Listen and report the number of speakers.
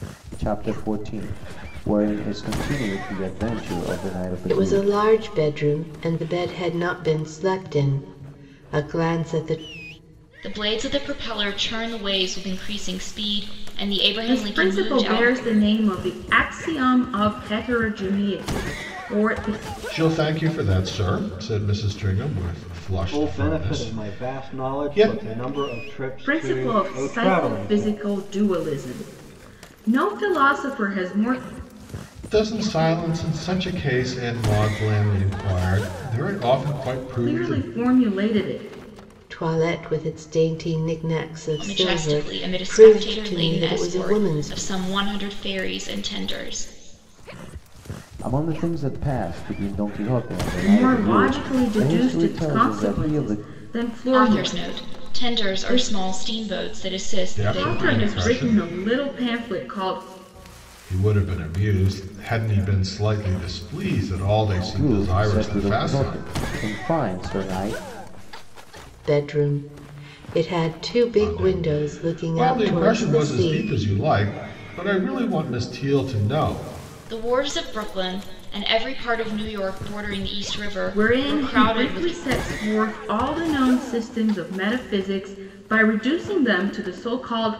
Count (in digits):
6